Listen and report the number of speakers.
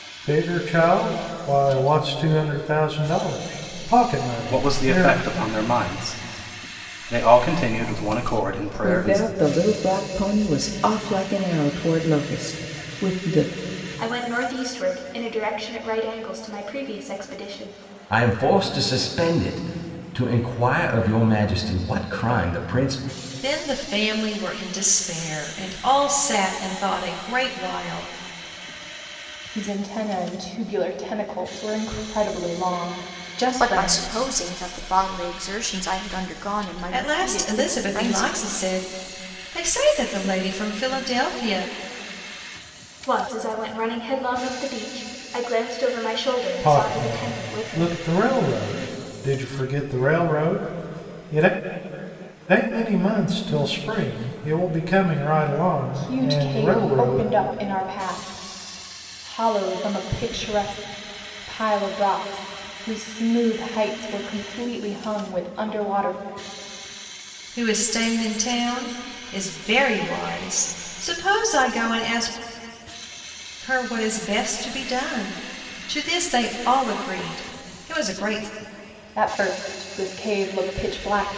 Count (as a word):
eight